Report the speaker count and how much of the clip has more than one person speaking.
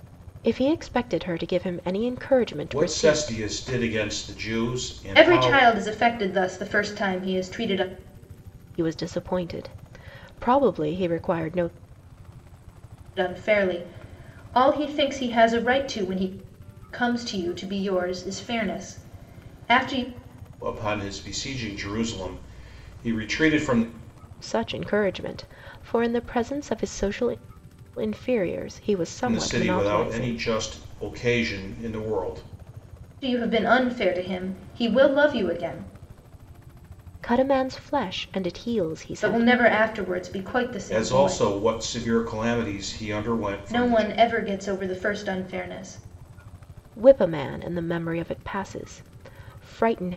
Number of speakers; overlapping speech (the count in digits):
3, about 8%